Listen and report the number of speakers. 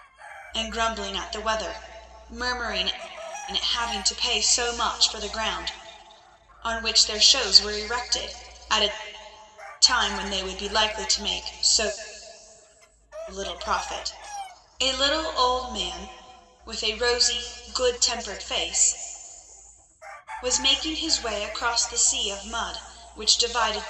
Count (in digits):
1